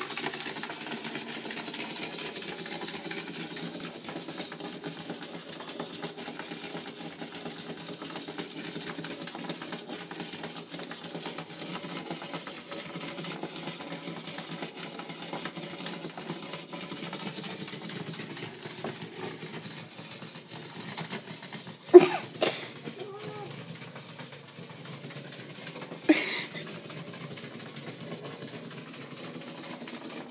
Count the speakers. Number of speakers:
0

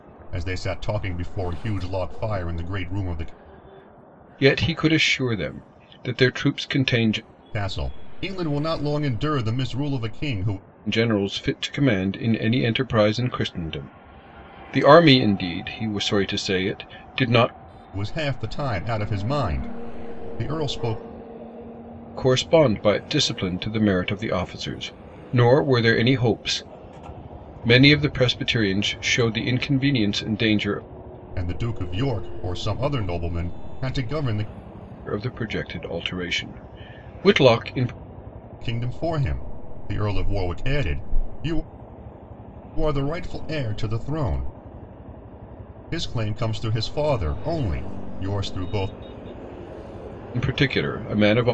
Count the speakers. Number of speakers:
2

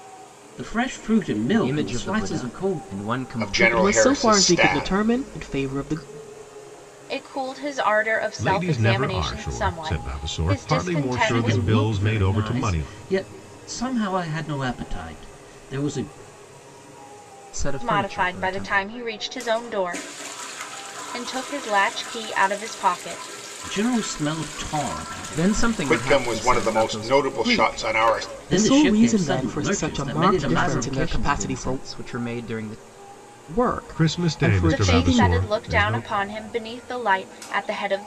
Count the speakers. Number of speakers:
6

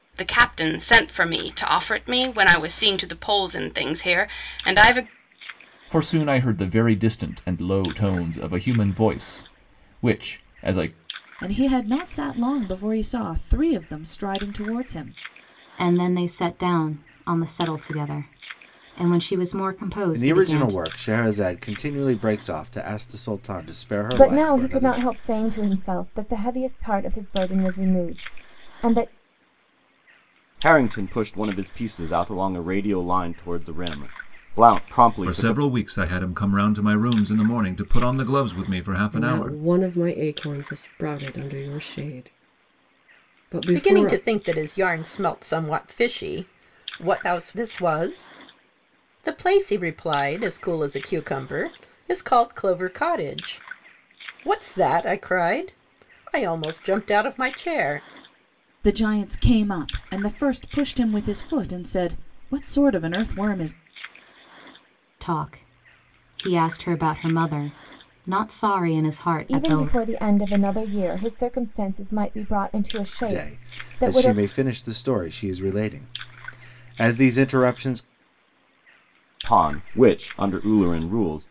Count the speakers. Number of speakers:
10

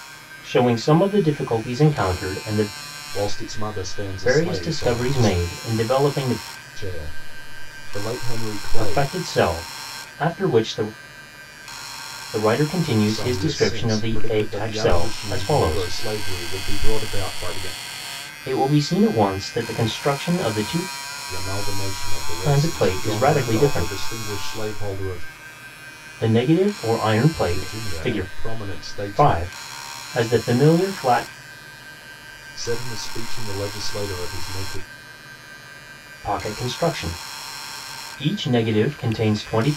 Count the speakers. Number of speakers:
2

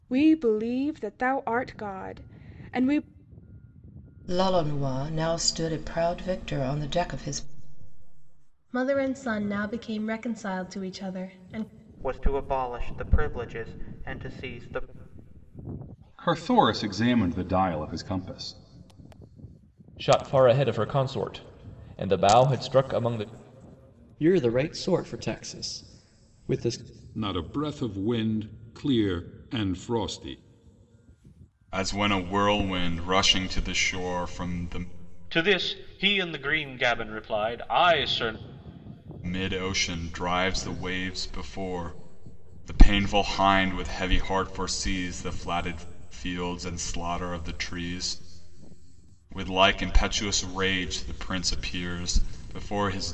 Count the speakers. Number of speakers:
10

